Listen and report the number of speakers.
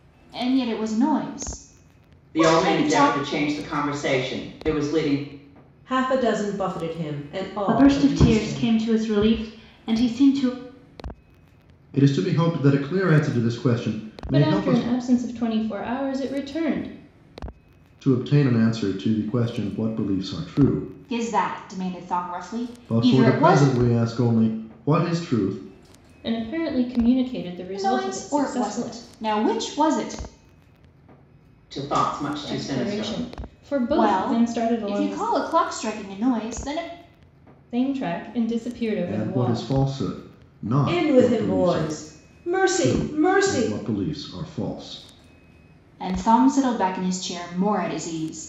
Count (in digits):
6